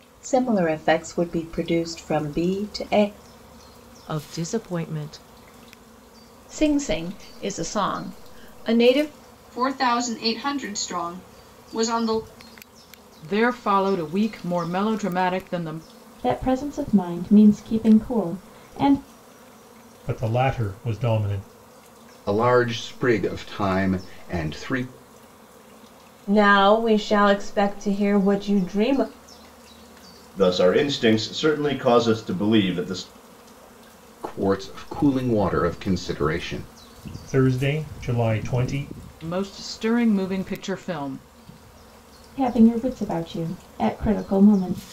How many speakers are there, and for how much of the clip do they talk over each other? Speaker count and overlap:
10, no overlap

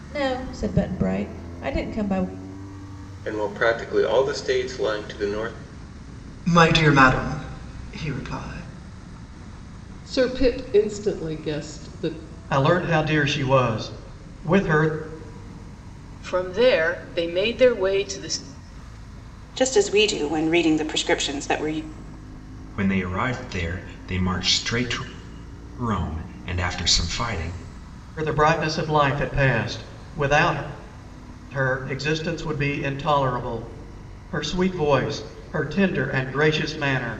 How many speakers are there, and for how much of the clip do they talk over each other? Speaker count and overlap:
8, no overlap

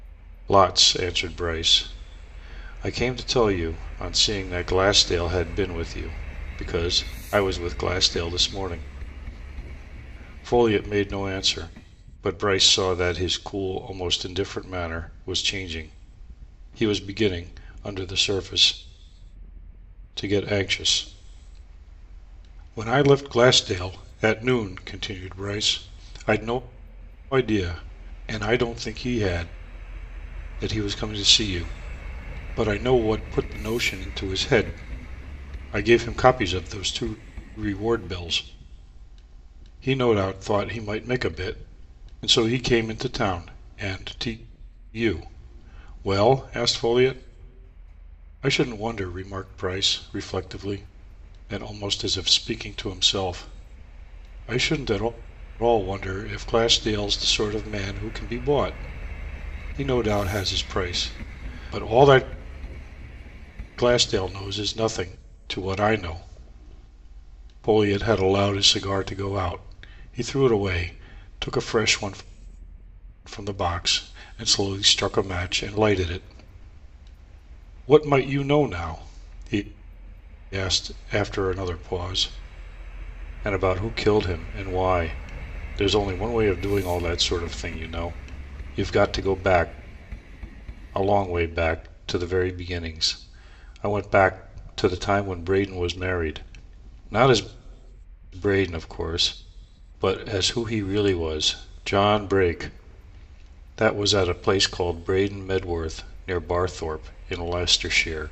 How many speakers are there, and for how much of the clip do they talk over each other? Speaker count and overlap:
1, no overlap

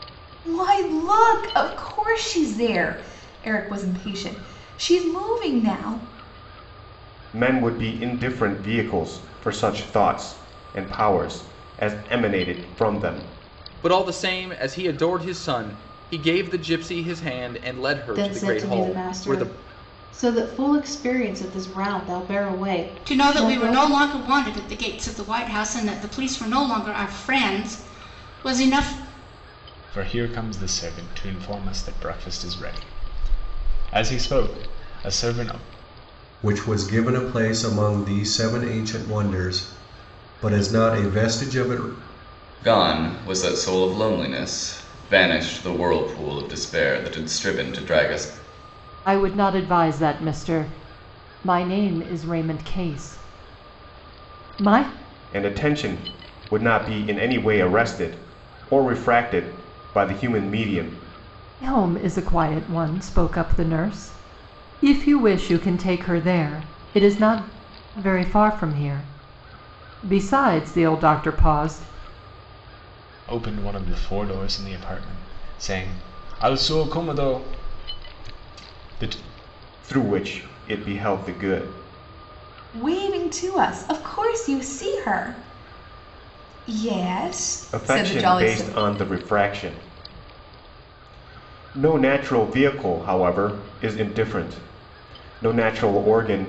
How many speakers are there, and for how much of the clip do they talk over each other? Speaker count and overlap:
9, about 4%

